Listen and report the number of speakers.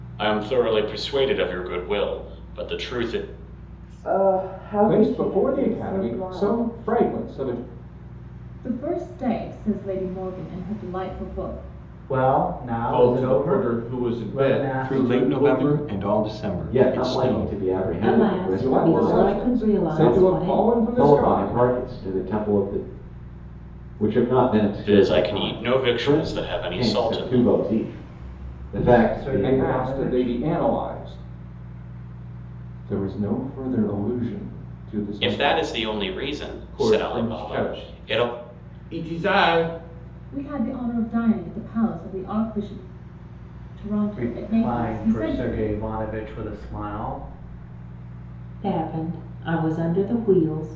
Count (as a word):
nine